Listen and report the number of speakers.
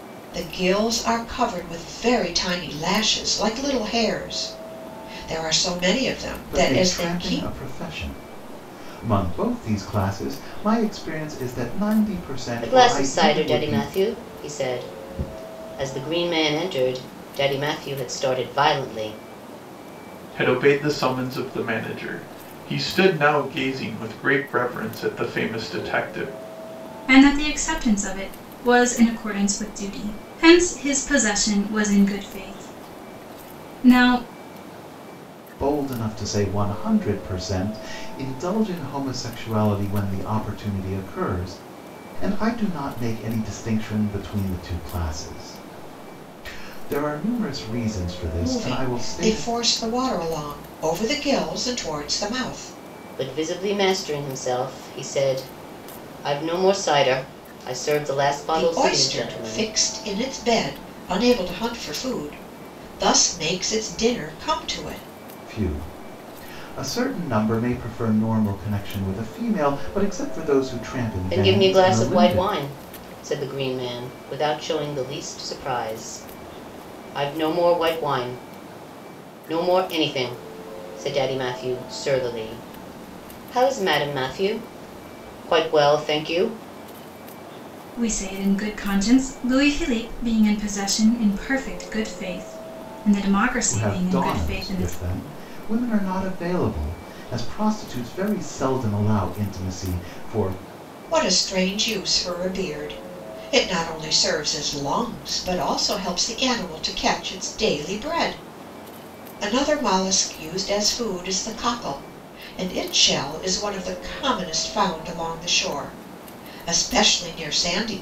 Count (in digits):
5